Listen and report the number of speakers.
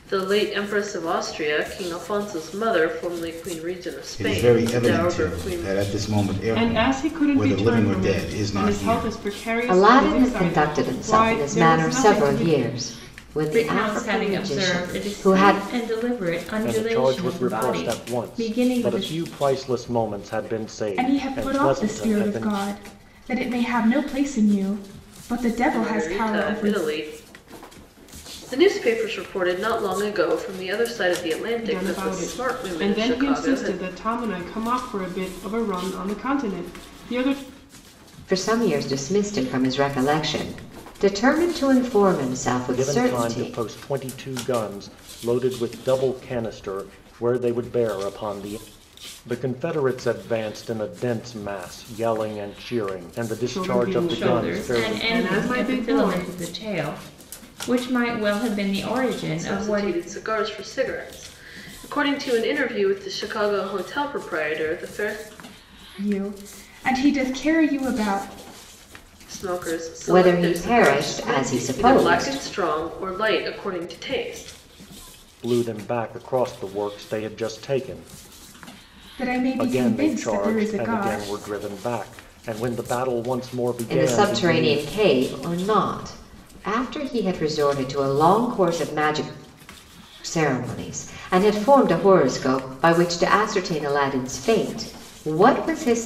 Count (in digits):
7